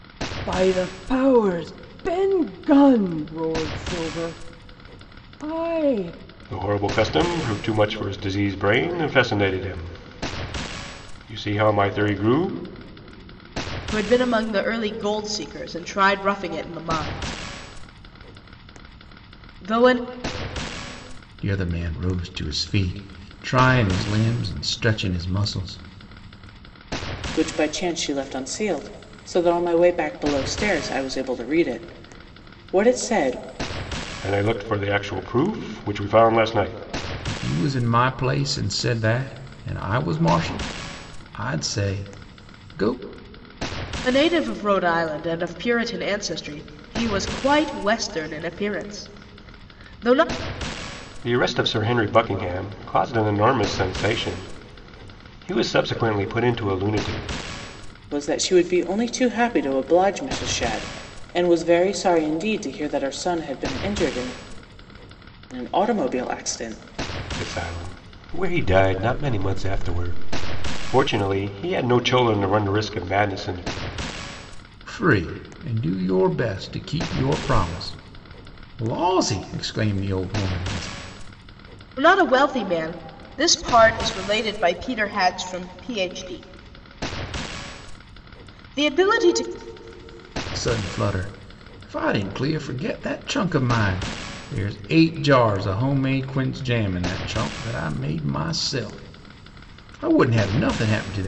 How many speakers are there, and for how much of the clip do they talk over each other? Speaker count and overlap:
five, no overlap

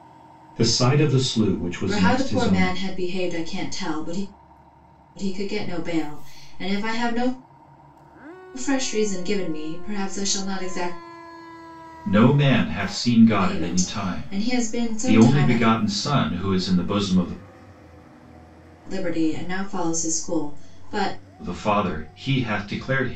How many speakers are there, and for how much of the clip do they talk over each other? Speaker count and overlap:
two, about 12%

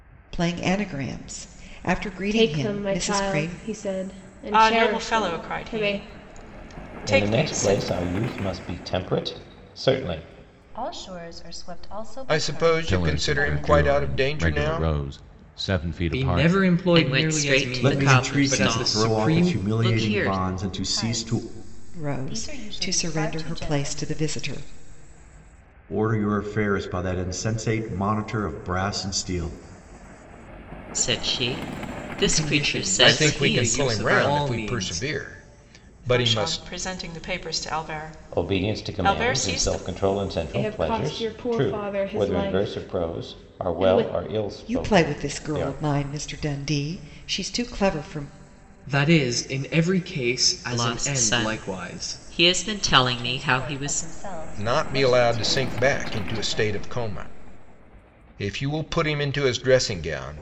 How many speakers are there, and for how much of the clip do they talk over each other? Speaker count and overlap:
ten, about 45%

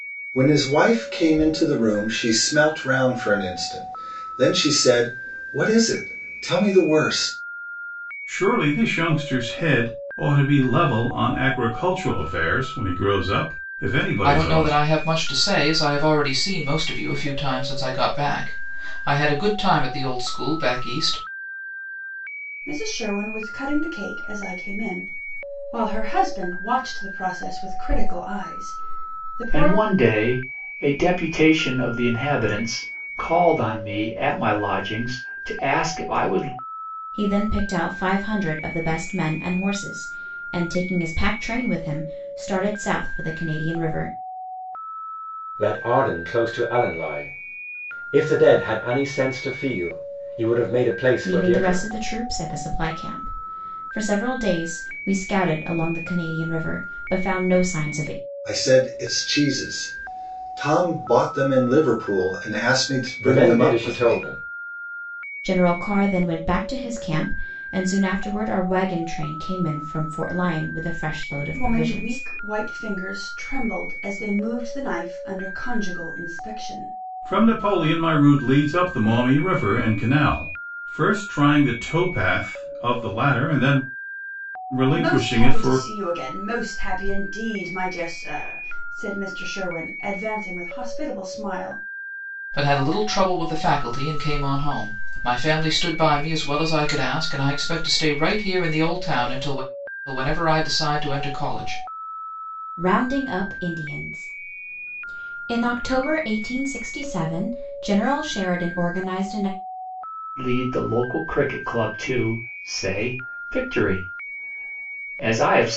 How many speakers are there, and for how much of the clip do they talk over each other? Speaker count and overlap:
seven, about 4%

